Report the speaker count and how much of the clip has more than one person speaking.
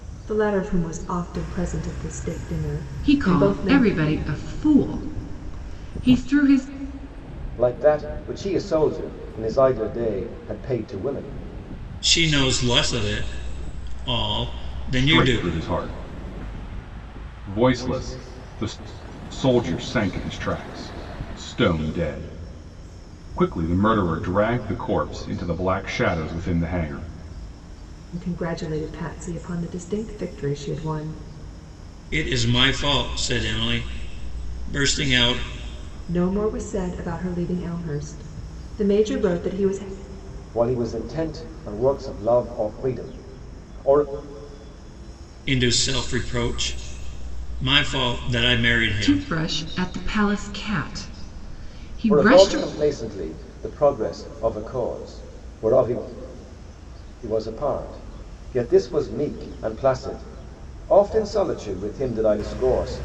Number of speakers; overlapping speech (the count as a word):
five, about 4%